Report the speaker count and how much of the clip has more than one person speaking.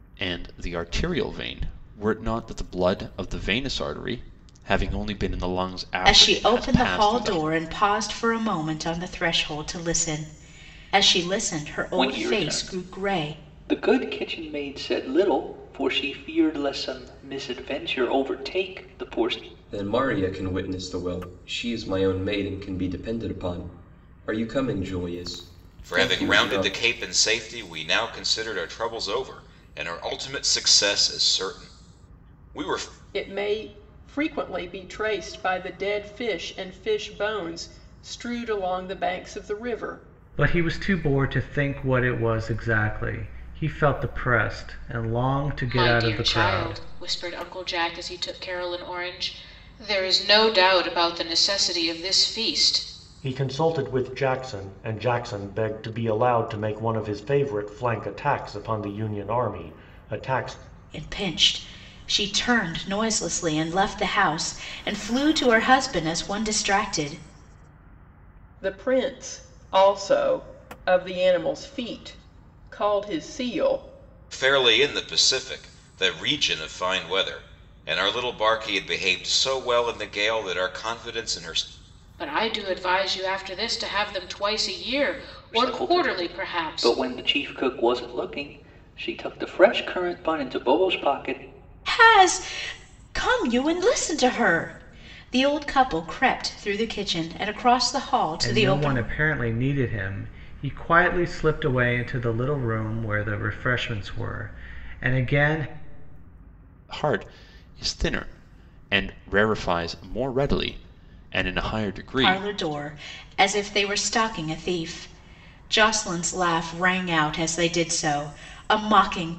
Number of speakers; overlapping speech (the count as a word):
nine, about 6%